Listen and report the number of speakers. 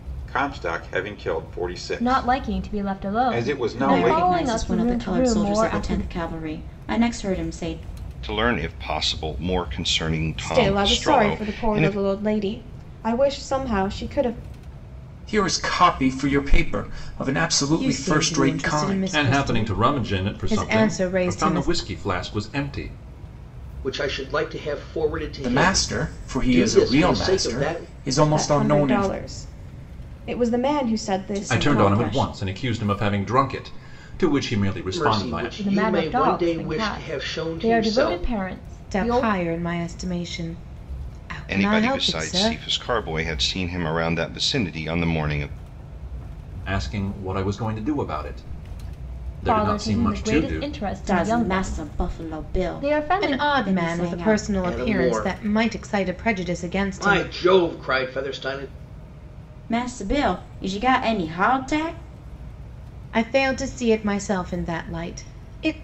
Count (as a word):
nine